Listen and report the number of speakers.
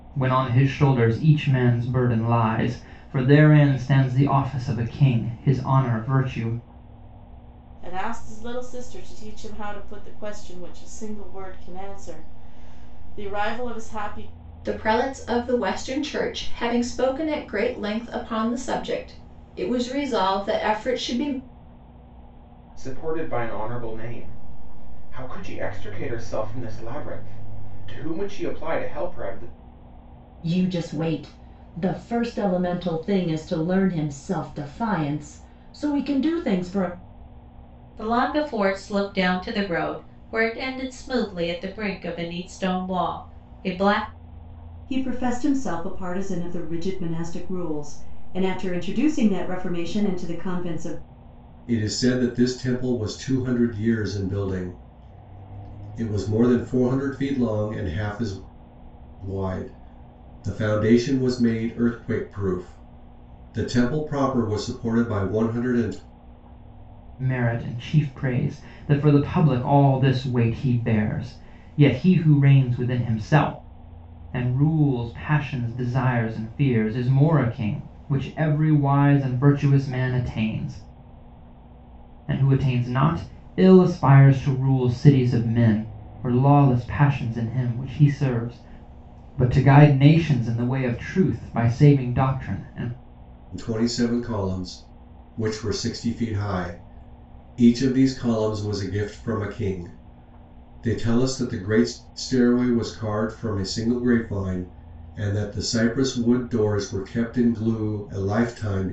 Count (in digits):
8